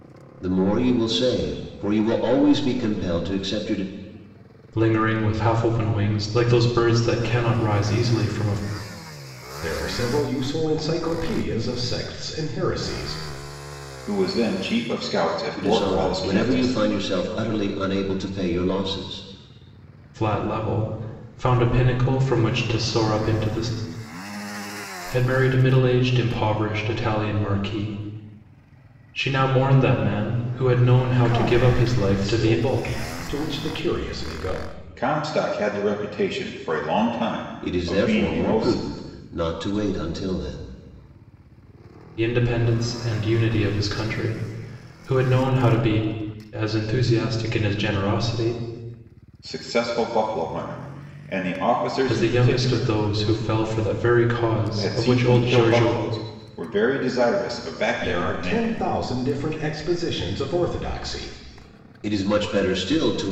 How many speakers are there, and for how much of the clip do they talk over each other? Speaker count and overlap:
four, about 11%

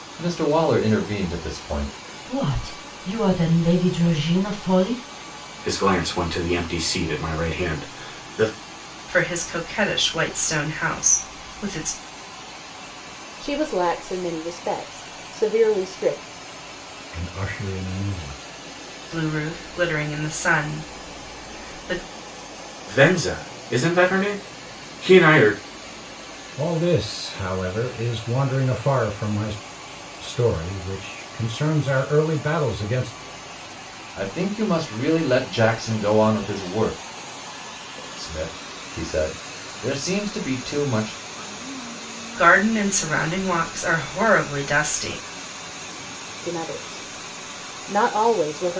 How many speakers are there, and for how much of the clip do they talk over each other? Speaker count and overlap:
six, no overlap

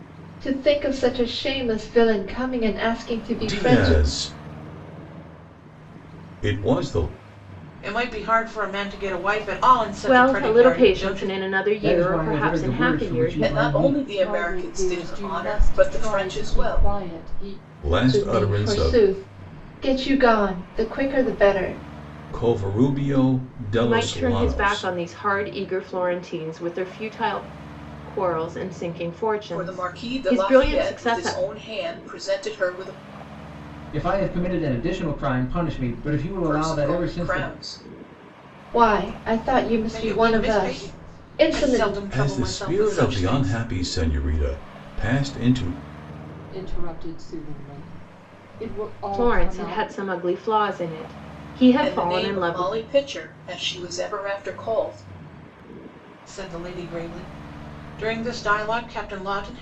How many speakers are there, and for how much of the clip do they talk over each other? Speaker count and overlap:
seven, about 29%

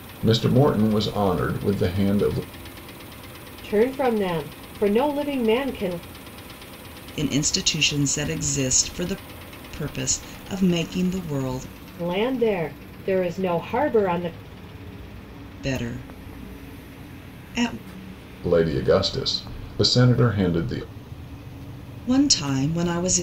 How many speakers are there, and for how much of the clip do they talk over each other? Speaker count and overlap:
three, no overlap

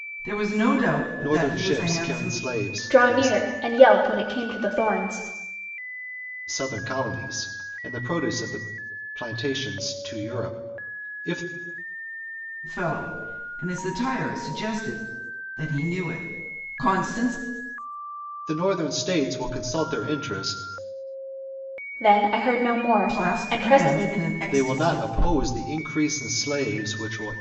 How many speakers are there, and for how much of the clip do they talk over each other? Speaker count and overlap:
three, about 13%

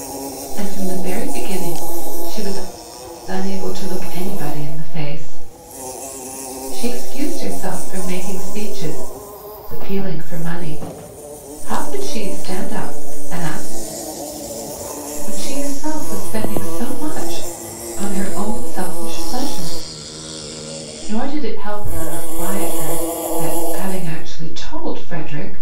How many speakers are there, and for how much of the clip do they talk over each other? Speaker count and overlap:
one, no overlap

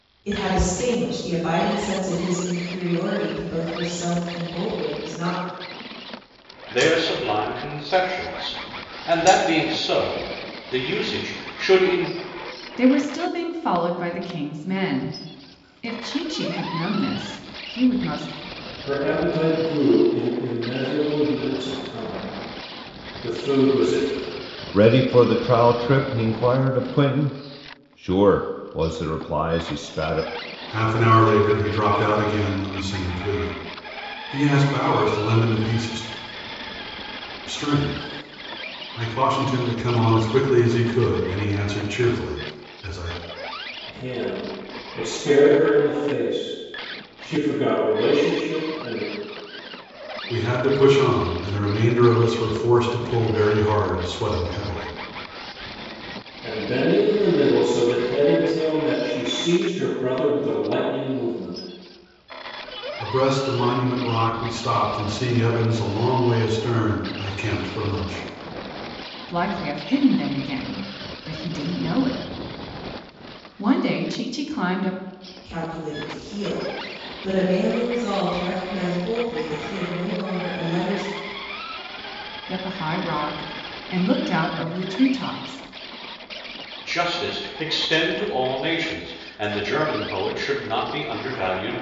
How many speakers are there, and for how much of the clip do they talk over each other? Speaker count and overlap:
six, no overlap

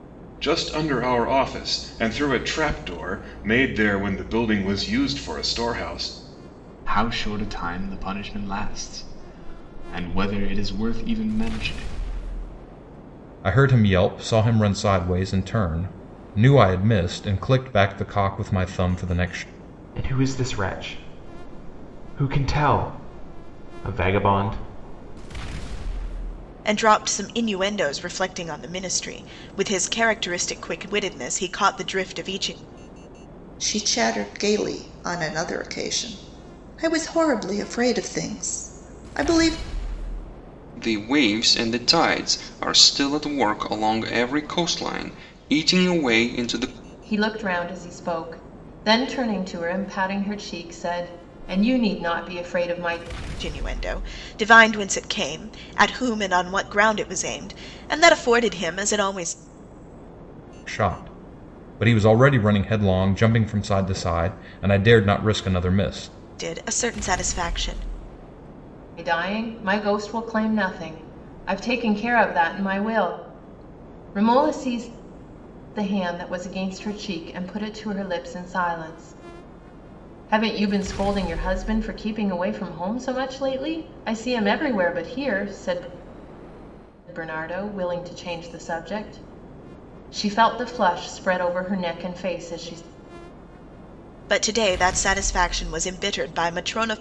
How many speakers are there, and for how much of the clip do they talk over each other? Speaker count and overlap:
eight, no overlap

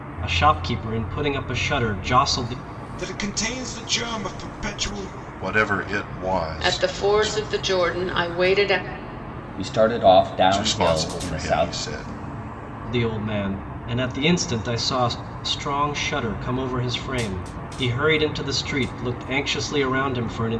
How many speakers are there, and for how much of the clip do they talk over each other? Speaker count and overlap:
five, about 10%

